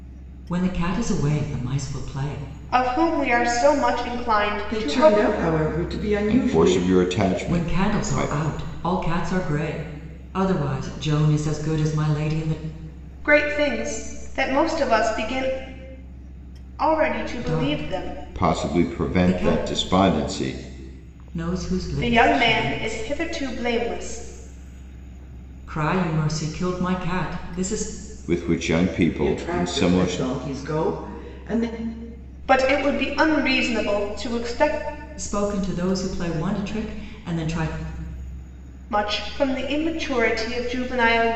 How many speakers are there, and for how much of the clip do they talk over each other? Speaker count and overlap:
4, about 16%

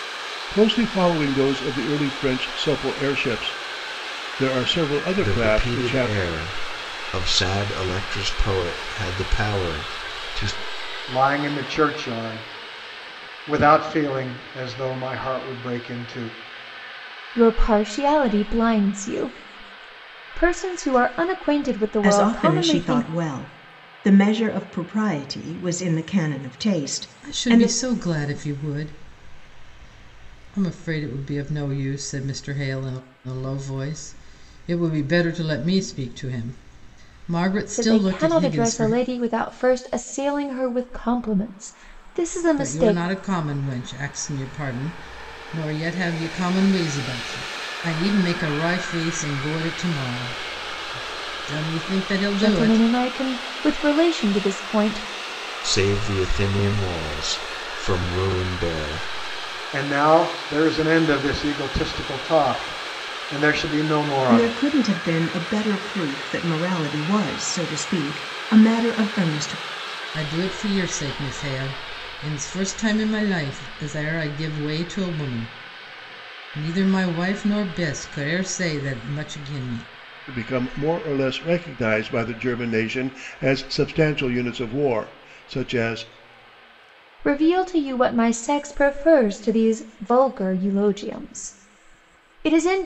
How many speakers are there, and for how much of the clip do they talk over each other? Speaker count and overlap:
6, about 6%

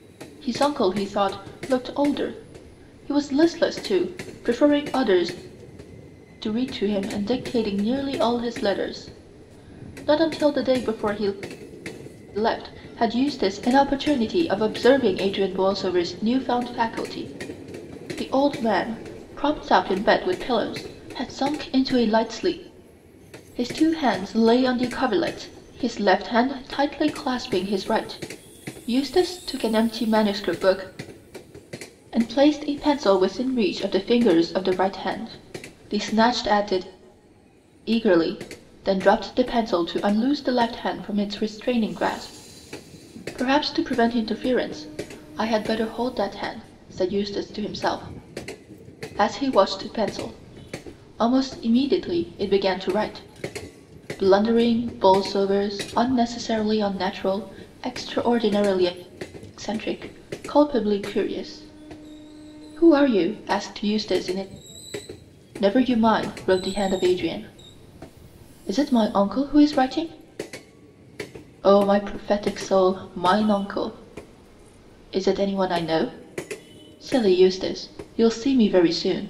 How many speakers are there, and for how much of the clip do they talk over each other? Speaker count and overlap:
1, no overlap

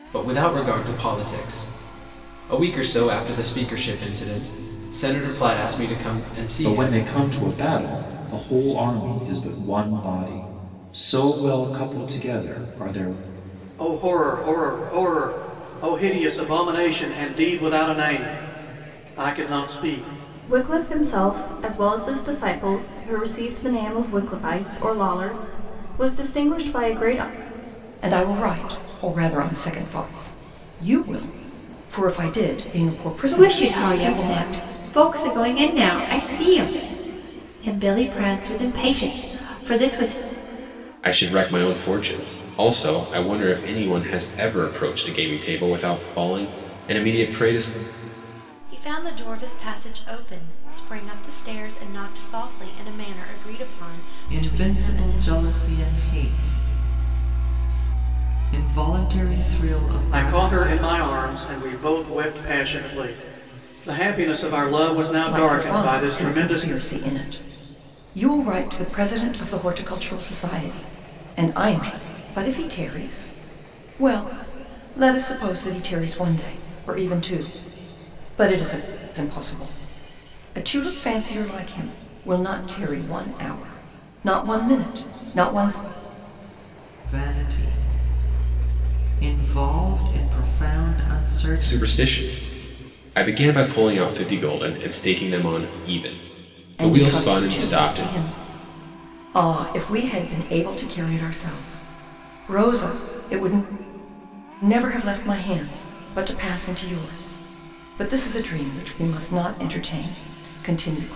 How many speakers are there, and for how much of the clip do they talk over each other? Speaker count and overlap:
9, about 6%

